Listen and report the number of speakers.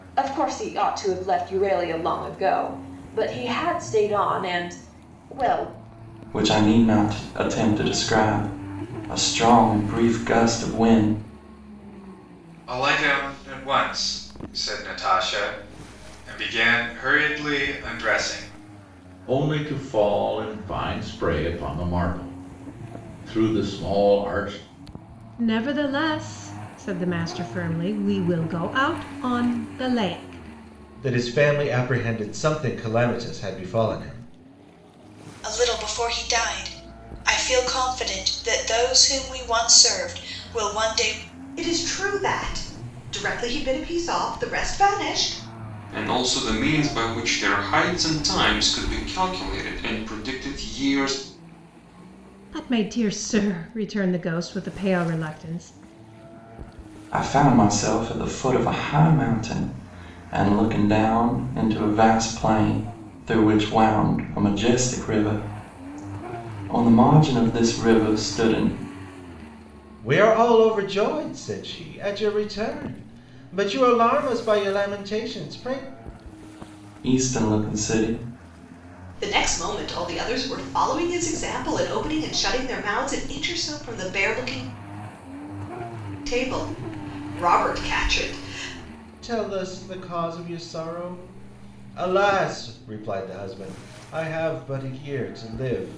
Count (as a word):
nine